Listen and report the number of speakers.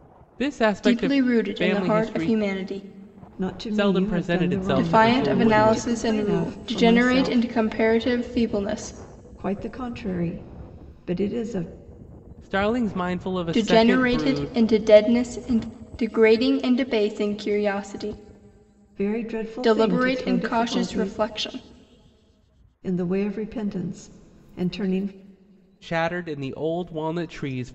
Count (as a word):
three